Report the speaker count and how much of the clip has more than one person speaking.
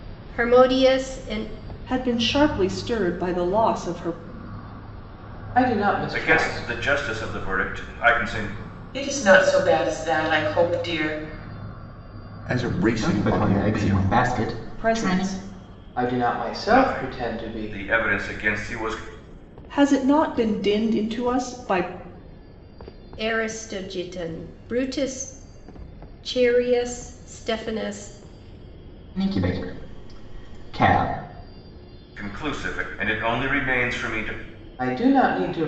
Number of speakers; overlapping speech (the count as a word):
seven, about 10%